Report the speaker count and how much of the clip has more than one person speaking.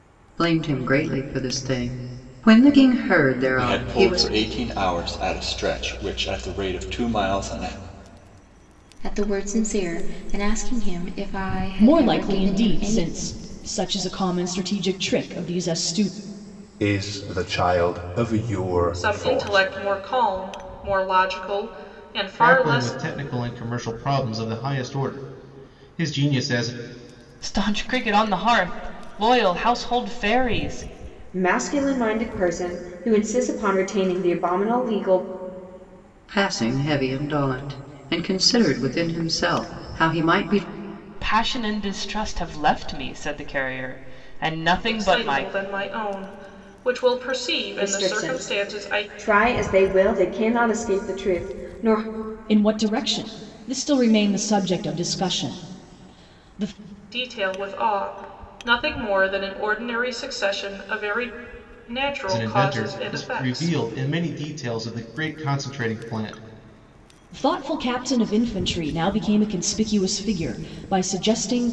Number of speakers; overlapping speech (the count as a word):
nine, about 10%